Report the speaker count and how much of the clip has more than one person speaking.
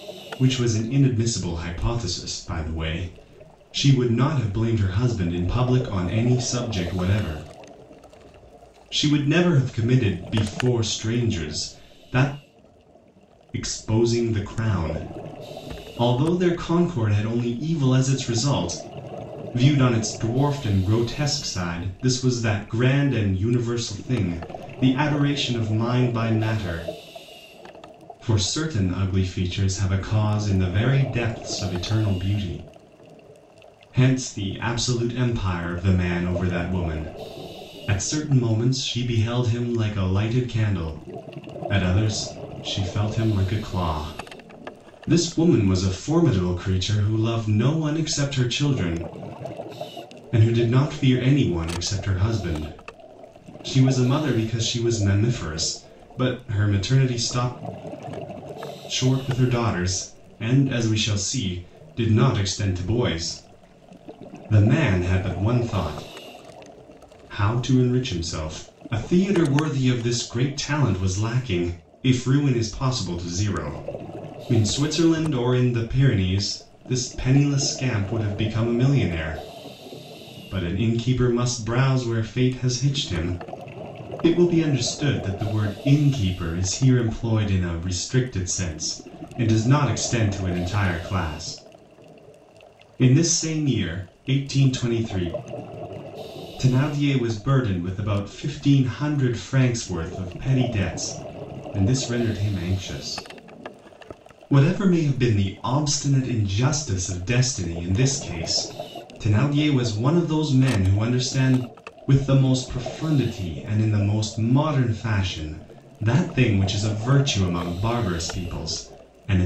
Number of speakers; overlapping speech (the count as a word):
one, no overlap